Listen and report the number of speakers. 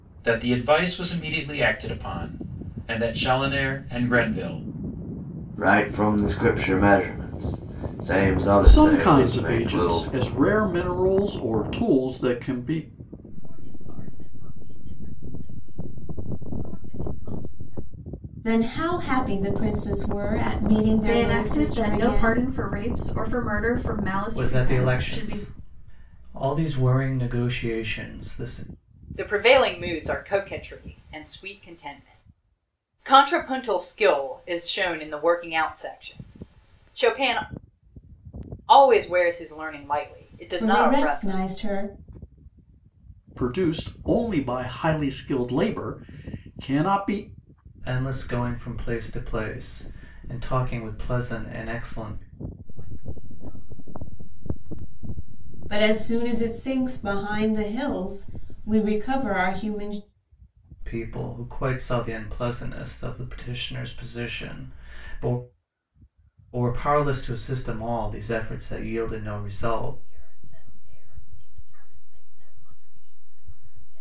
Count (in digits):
8